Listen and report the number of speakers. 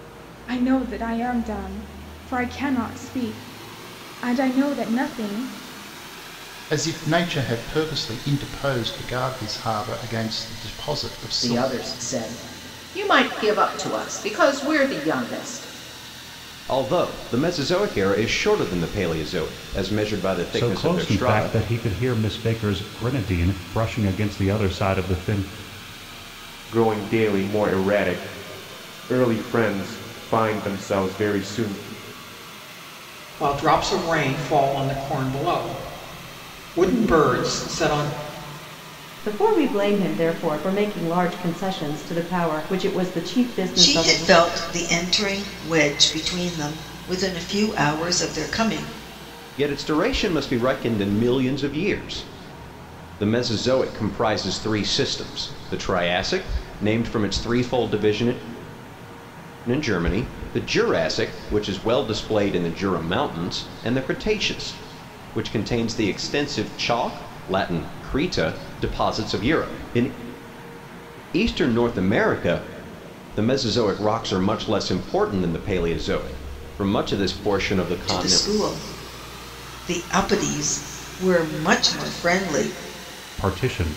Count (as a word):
nine